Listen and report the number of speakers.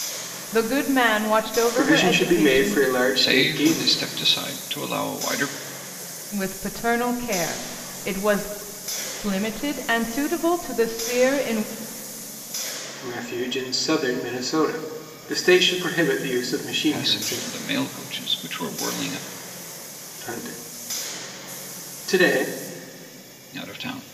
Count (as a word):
three